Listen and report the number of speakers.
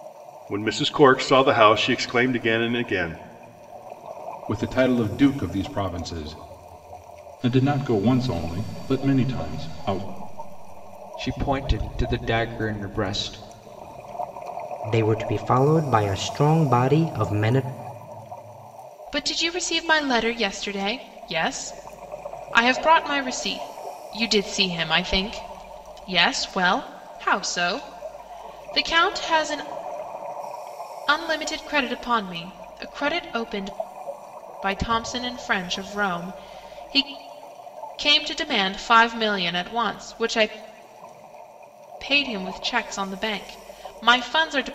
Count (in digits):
6